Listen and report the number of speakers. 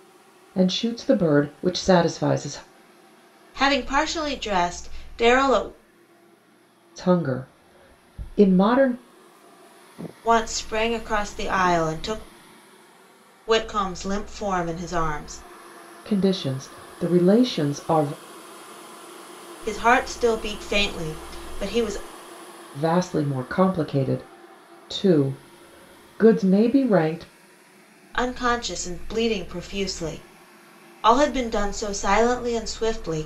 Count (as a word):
two